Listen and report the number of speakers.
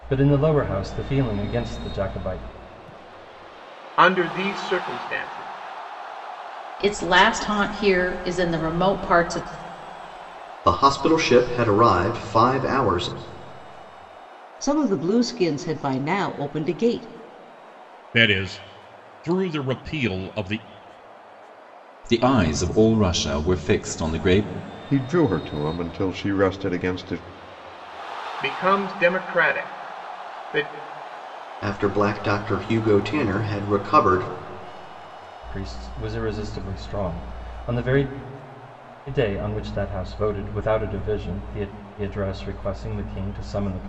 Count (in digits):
8